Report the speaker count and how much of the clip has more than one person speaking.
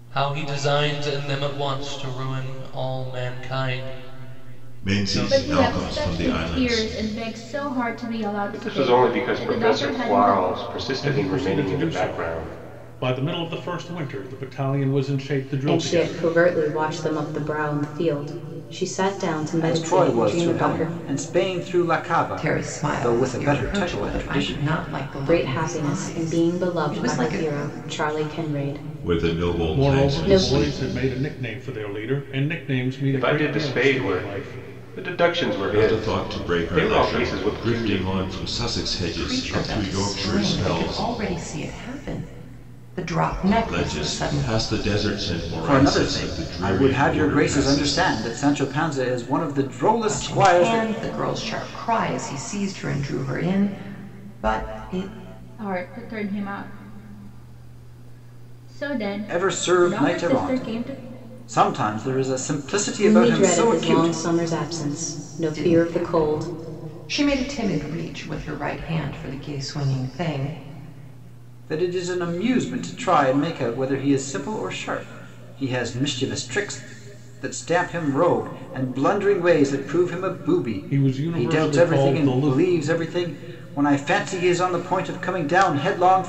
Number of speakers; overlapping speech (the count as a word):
eight, about 35%